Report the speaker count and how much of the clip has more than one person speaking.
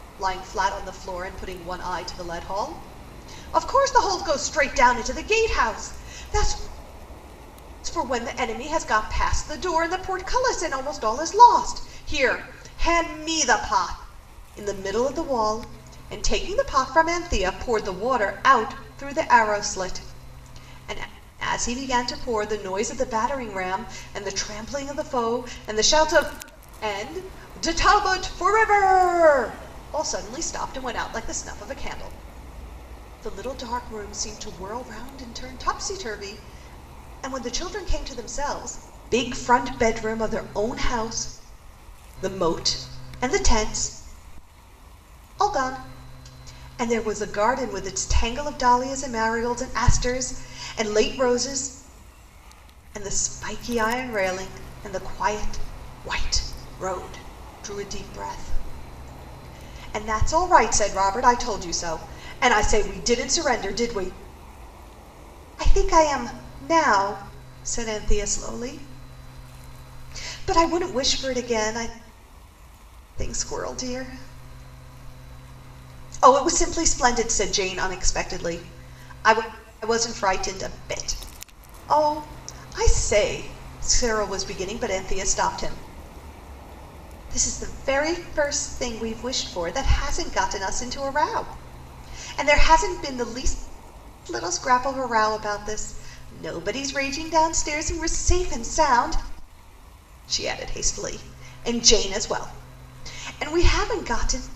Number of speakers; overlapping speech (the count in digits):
1, no overlap